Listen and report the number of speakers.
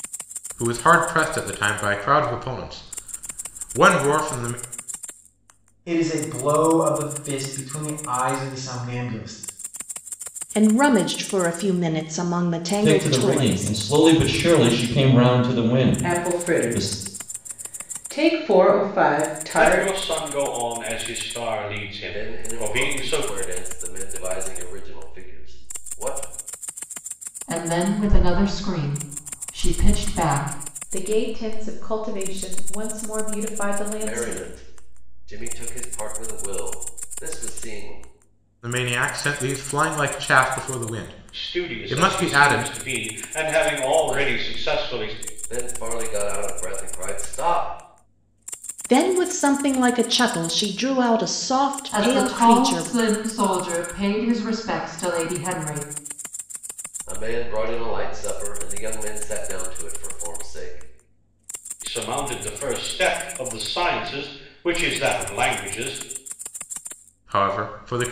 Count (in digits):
9